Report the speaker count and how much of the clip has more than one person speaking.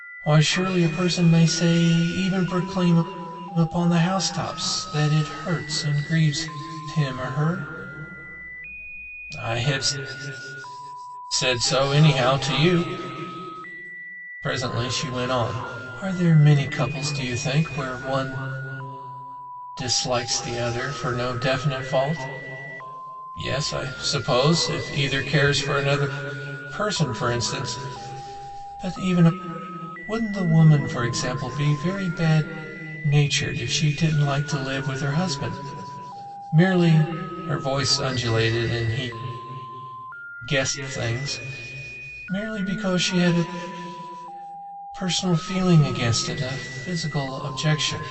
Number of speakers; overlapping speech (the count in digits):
1, no overlap